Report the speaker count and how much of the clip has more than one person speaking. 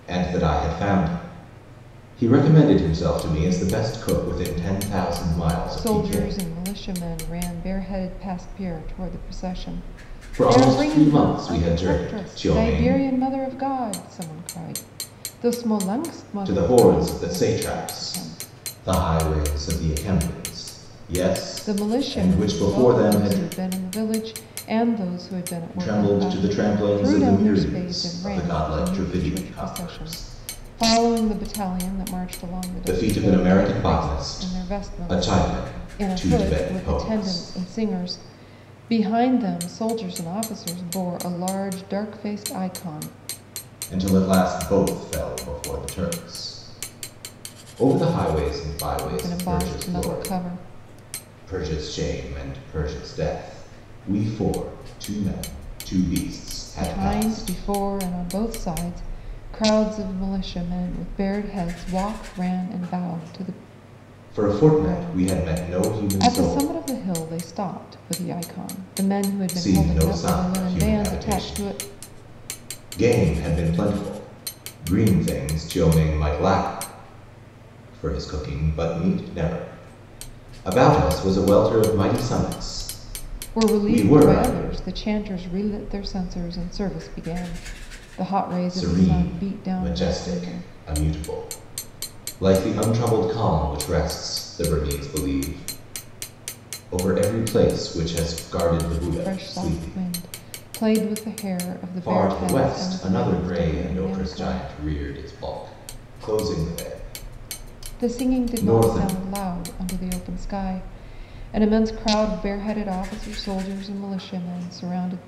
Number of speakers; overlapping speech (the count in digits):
2, about 26%